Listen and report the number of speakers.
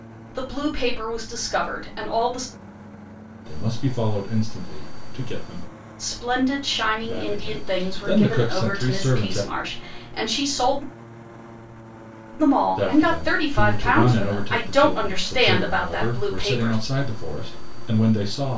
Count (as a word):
two